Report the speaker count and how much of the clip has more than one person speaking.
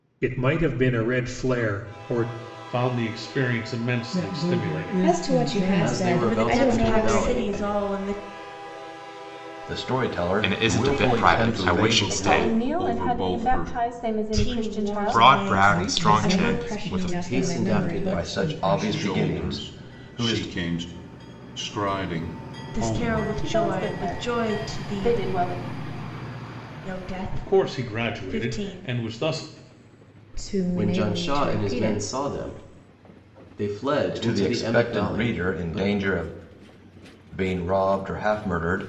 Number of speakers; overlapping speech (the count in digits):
10, about 53%